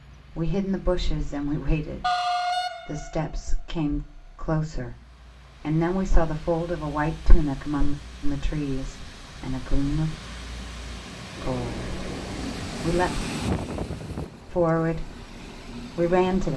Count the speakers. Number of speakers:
1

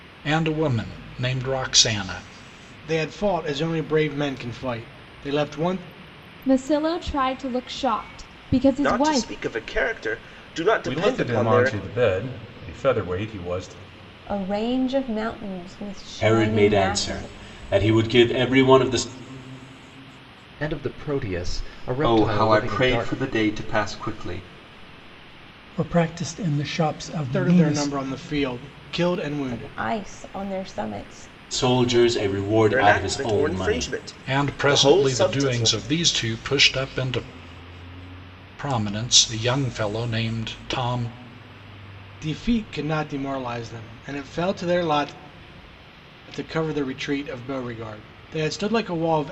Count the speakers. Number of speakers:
10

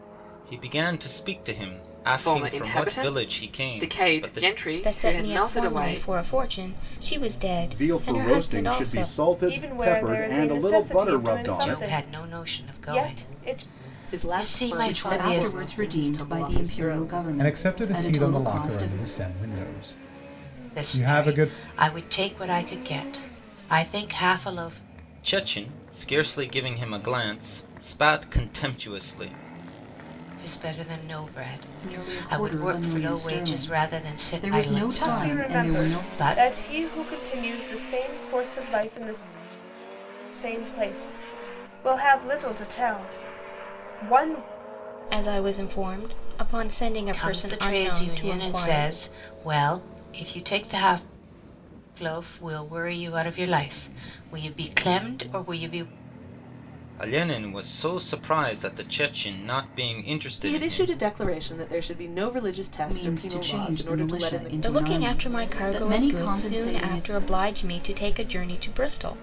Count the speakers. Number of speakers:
9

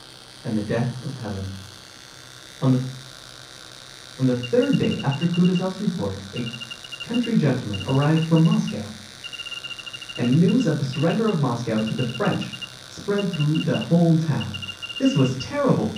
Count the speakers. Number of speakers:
1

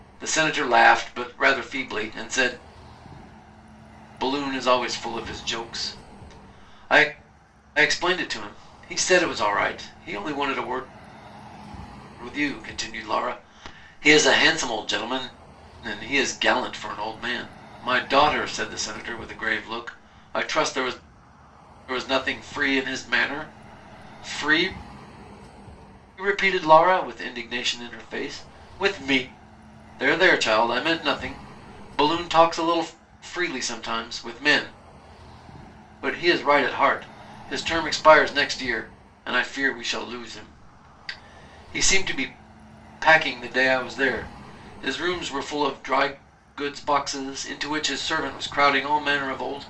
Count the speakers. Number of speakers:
1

